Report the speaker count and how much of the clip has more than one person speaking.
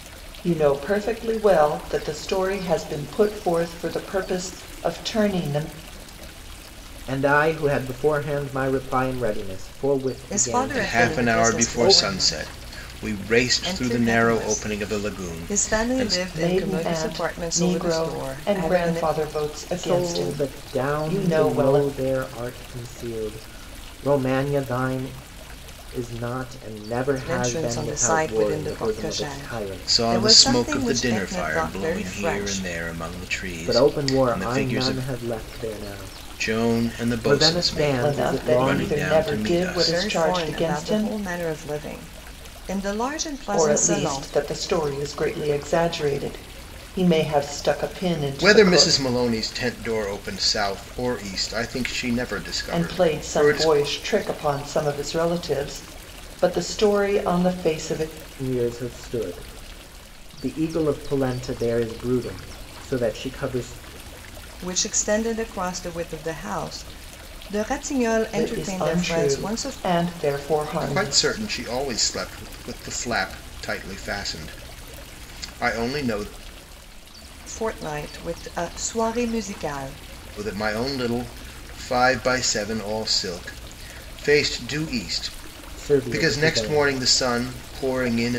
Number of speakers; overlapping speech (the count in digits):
4, about 30%